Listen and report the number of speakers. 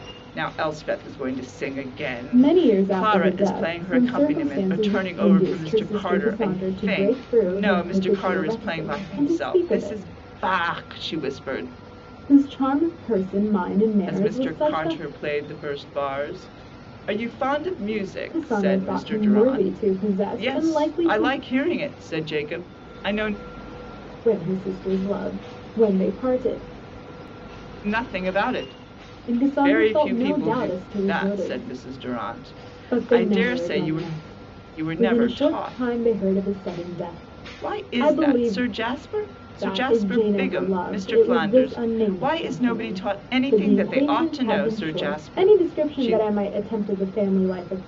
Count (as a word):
two